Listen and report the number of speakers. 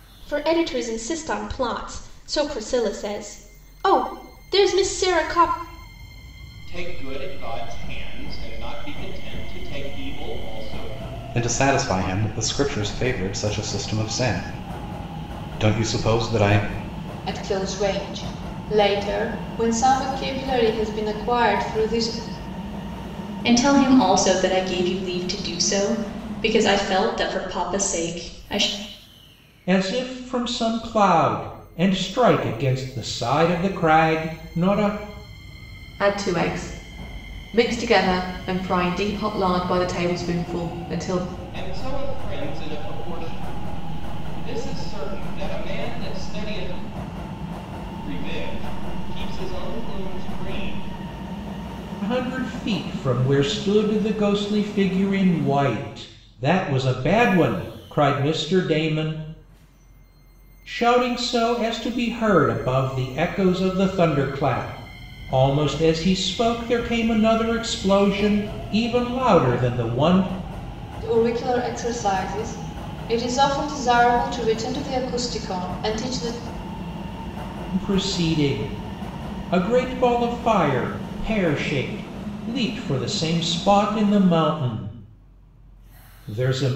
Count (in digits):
7